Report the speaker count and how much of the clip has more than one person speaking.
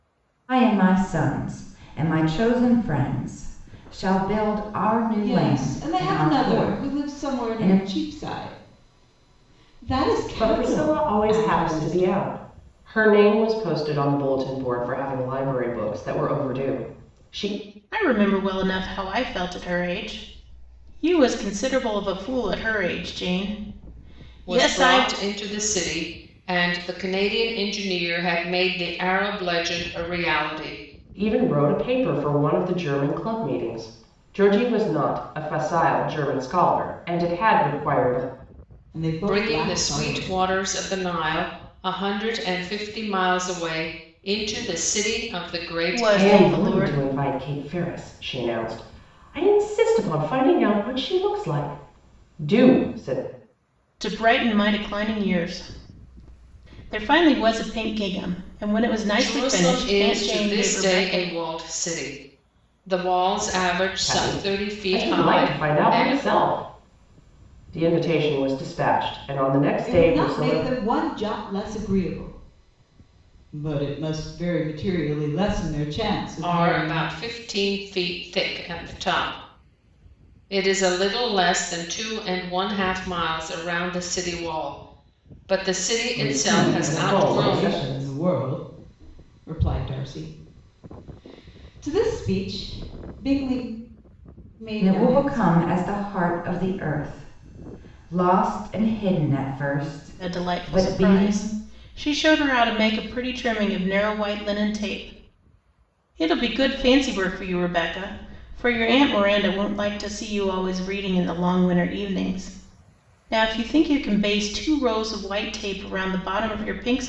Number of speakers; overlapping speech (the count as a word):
five, about 15%